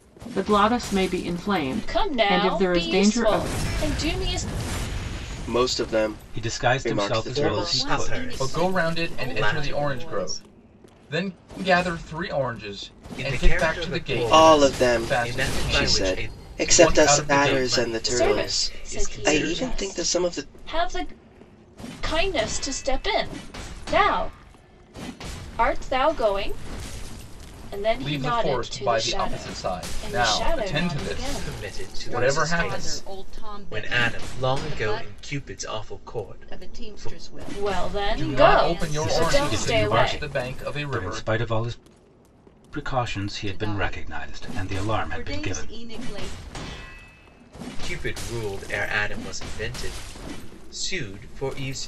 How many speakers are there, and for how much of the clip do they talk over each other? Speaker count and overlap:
7, about 52%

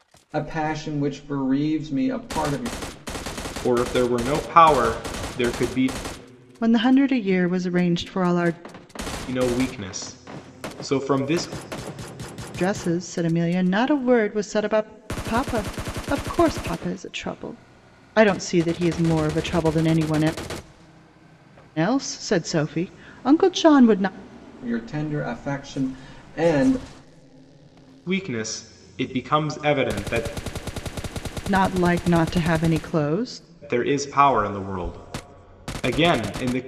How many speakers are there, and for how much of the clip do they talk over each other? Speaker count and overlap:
3, no overlap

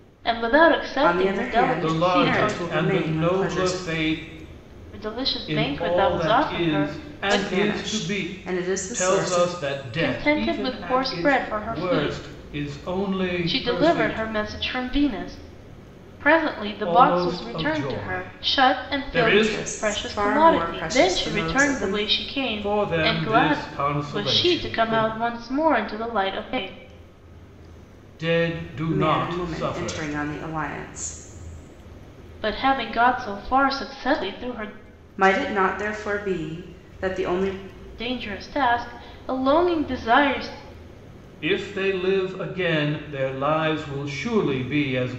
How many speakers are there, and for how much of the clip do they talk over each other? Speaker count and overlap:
3, about 39%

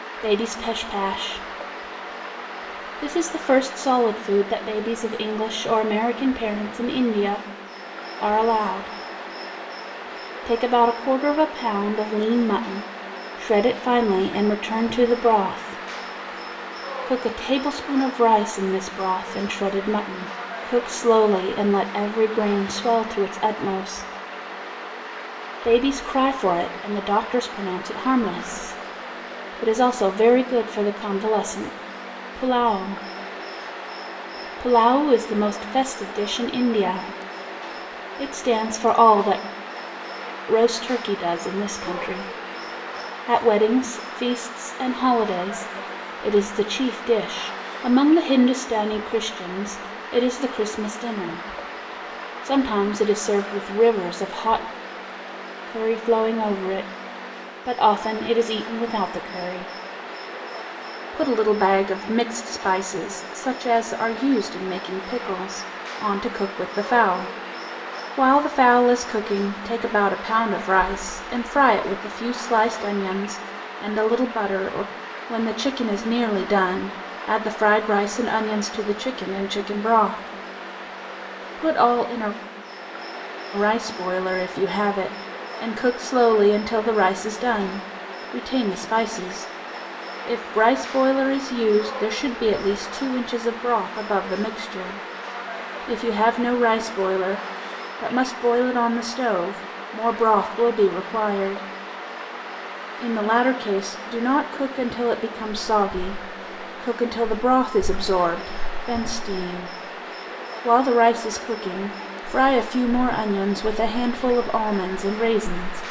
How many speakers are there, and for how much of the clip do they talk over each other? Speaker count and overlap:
1, no overlap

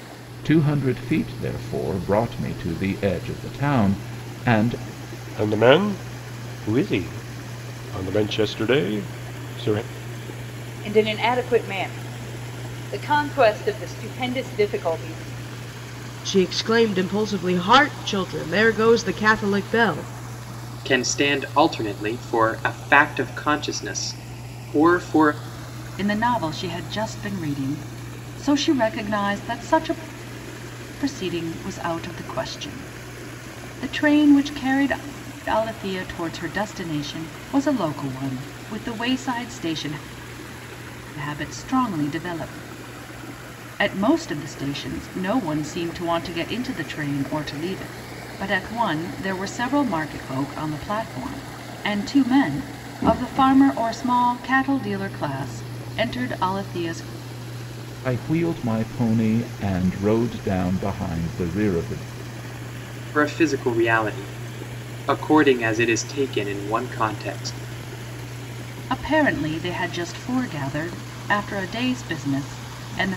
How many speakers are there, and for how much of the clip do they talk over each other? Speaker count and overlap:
6, no overlap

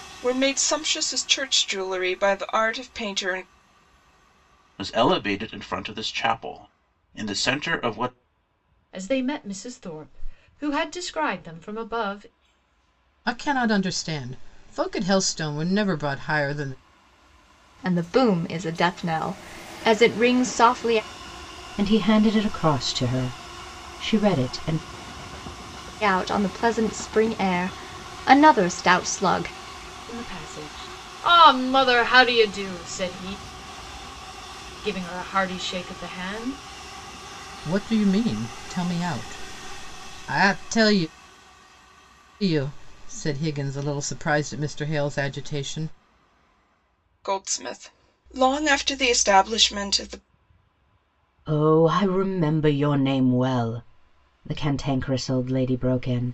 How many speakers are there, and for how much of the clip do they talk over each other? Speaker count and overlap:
6, no overlap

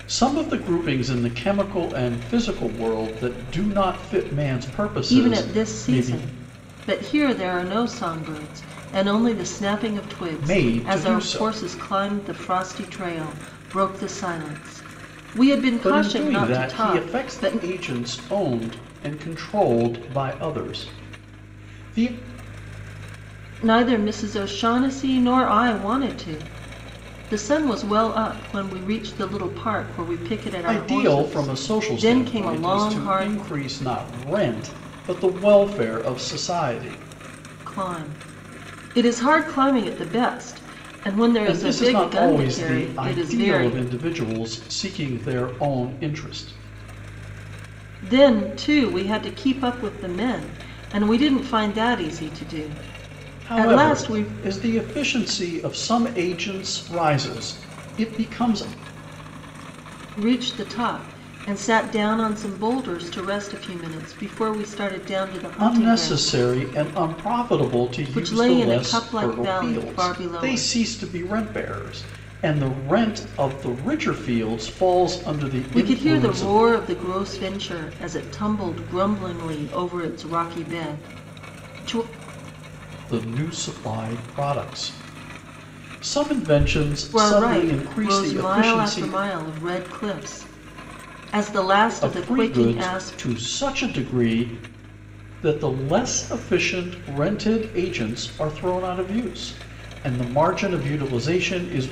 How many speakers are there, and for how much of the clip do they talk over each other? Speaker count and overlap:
2, about 17%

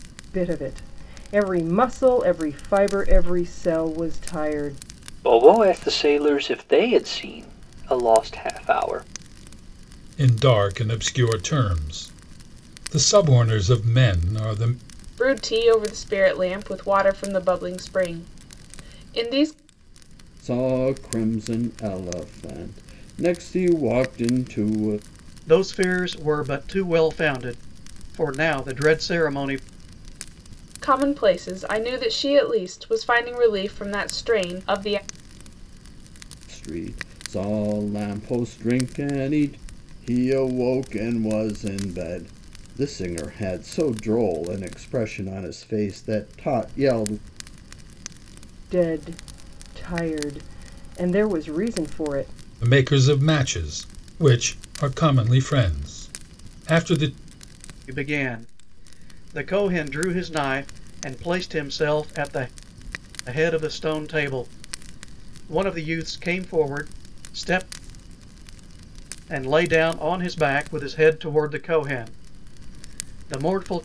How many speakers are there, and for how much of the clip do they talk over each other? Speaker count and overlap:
6, no overlap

